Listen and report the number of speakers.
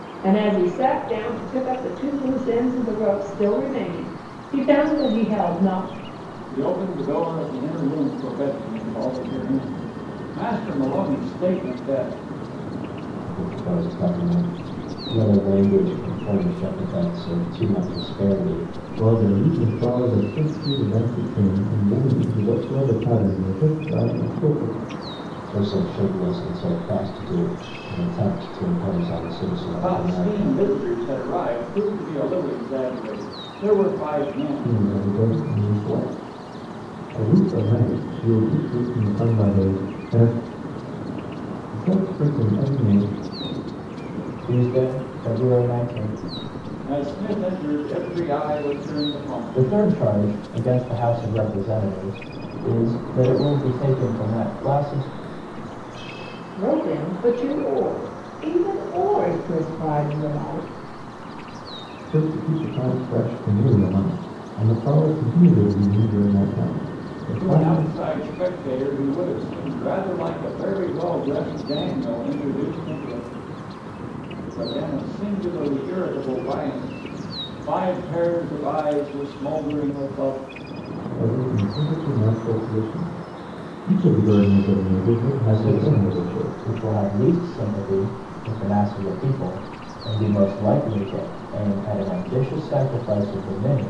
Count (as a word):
four